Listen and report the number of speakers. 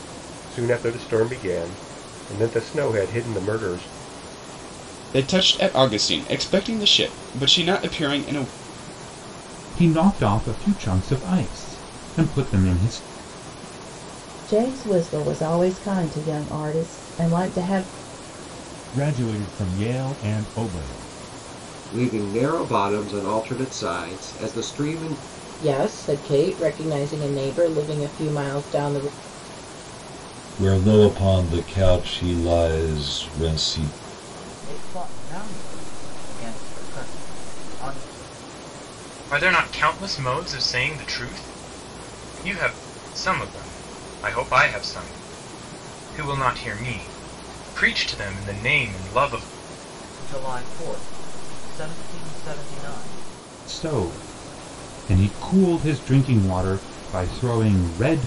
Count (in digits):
10